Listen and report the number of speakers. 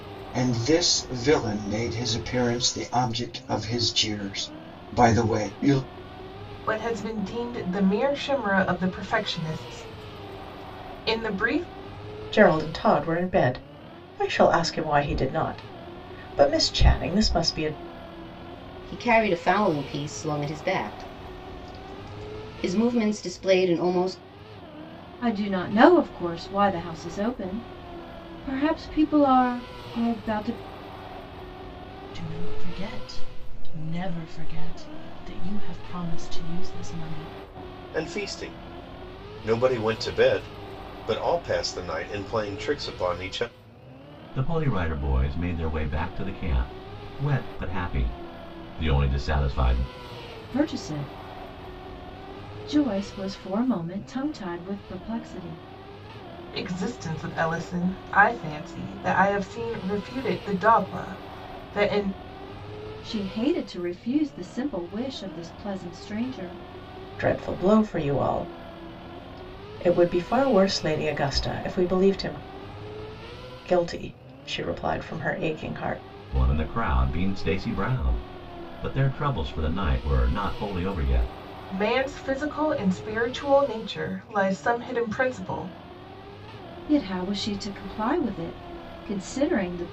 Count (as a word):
eight